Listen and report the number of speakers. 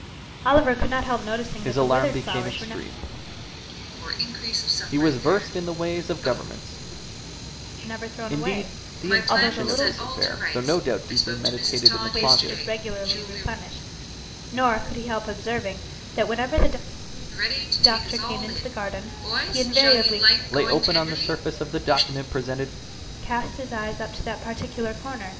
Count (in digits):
3